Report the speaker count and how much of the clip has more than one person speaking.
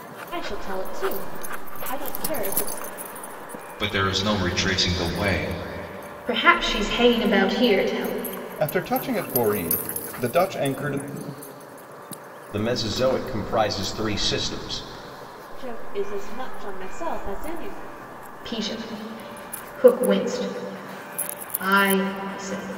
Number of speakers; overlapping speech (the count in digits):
5, no overlap